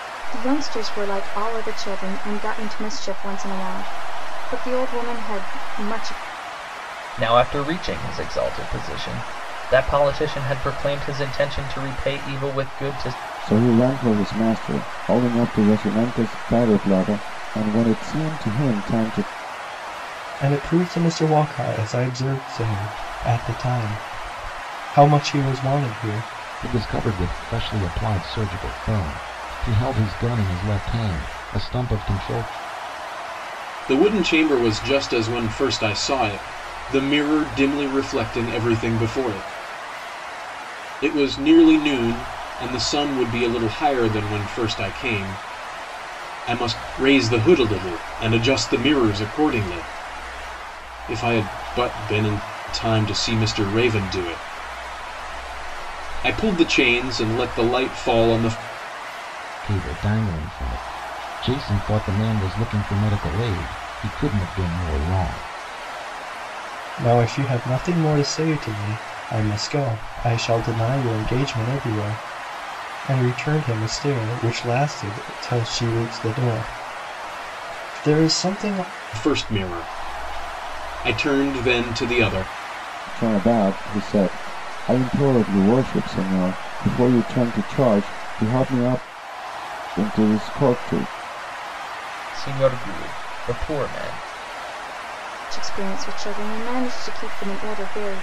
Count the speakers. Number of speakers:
6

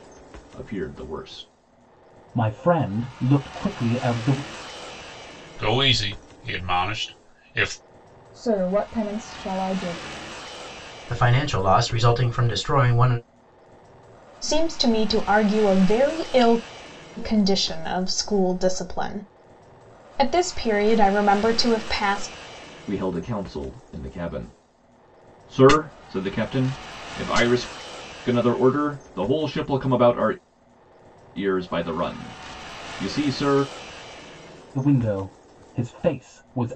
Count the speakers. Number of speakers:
6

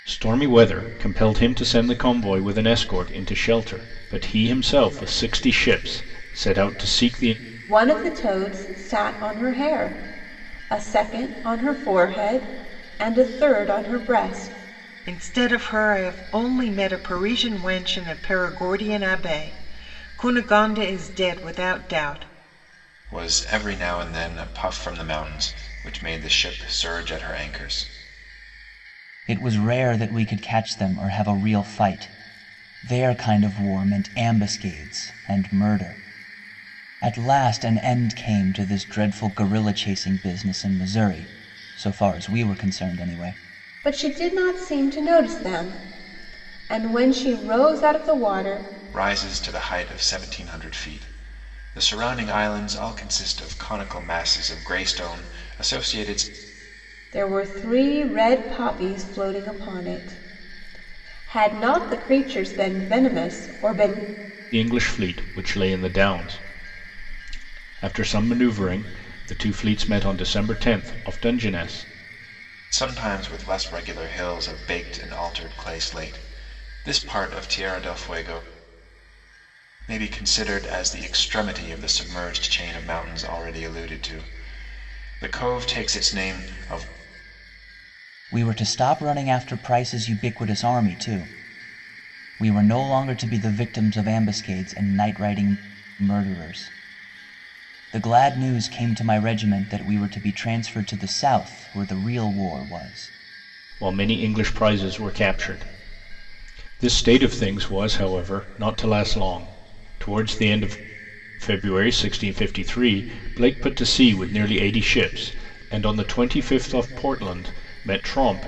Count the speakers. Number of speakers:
5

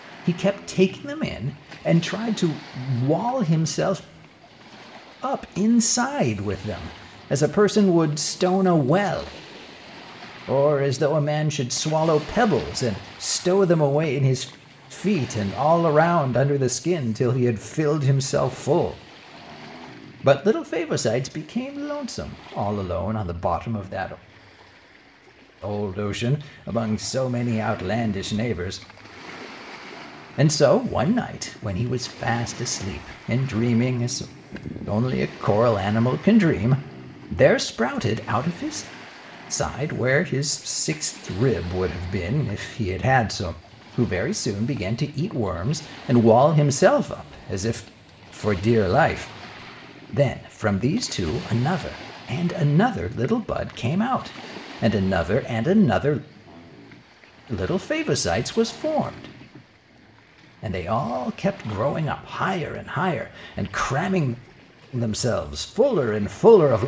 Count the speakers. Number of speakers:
1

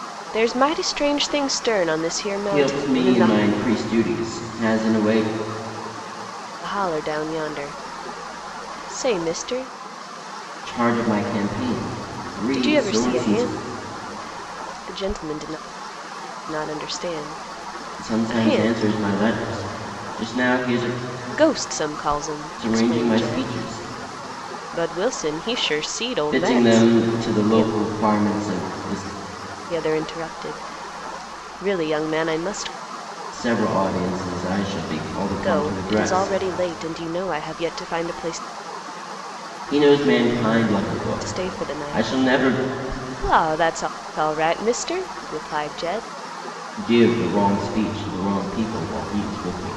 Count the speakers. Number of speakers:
2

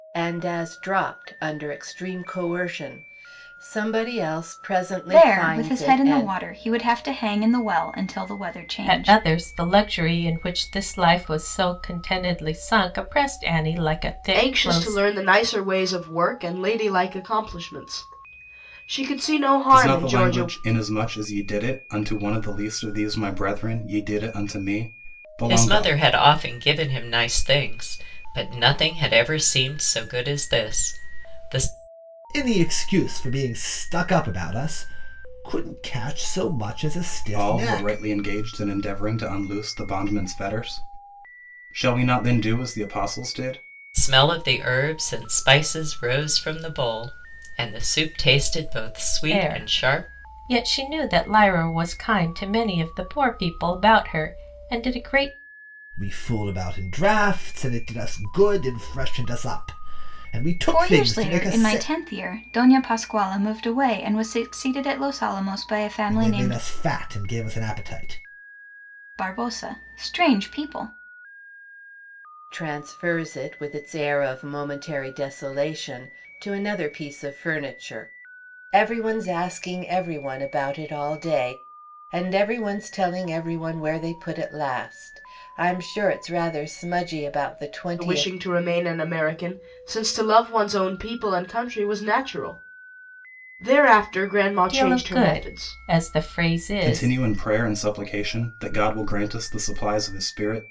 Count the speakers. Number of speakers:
7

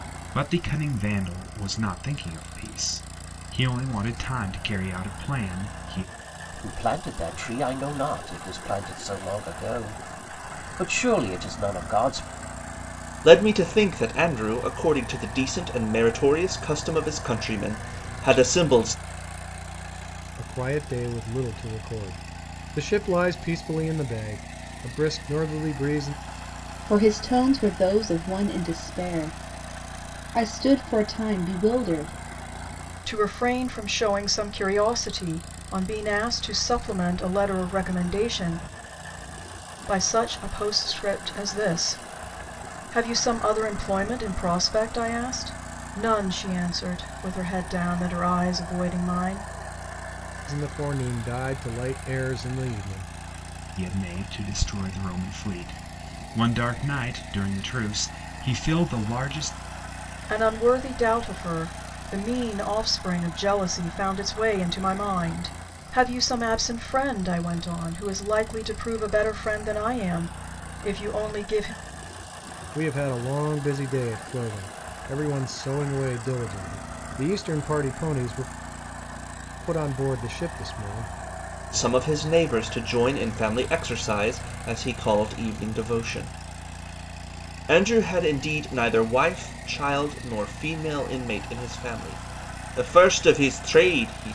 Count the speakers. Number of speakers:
6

